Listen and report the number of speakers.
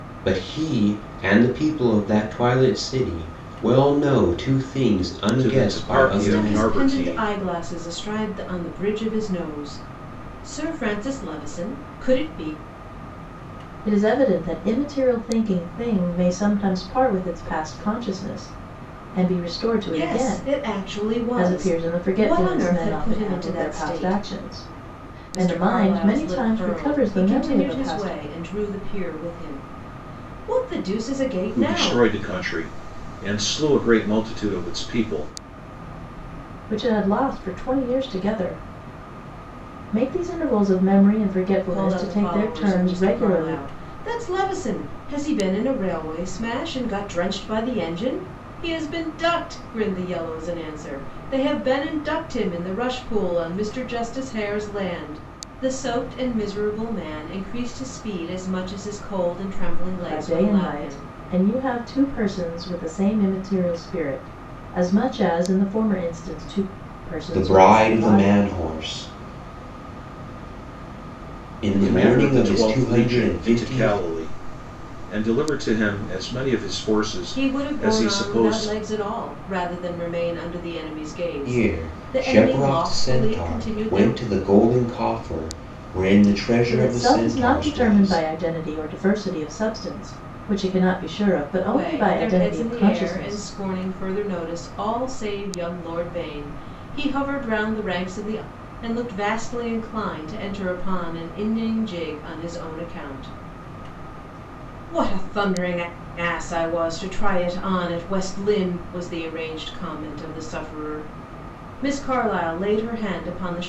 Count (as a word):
four